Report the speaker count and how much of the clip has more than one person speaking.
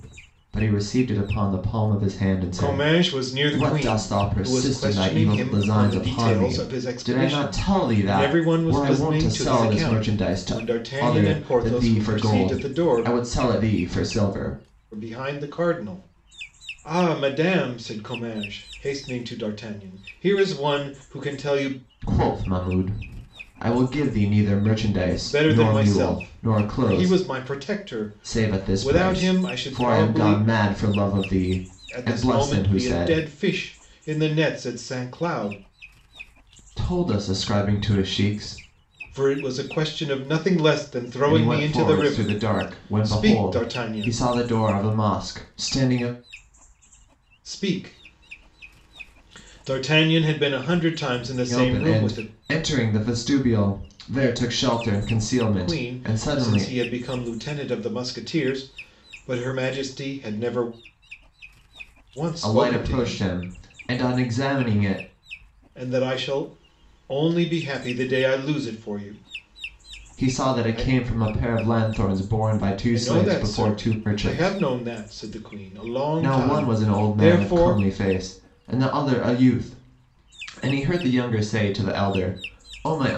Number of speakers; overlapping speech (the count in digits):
2, about 30%